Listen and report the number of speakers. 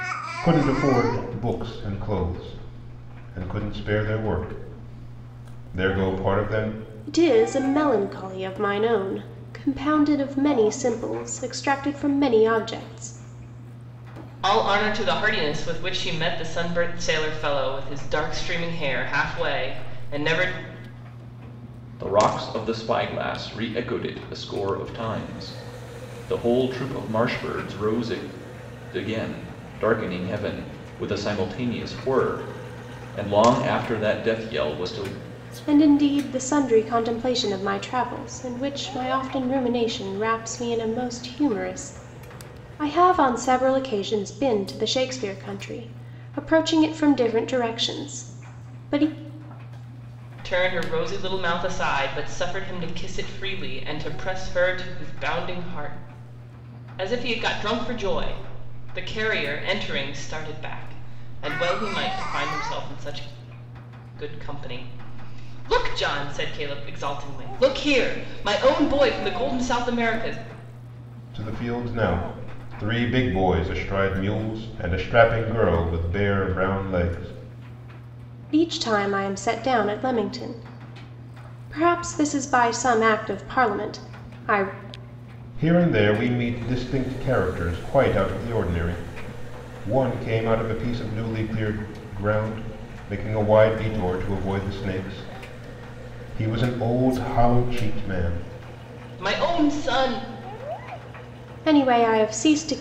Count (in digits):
4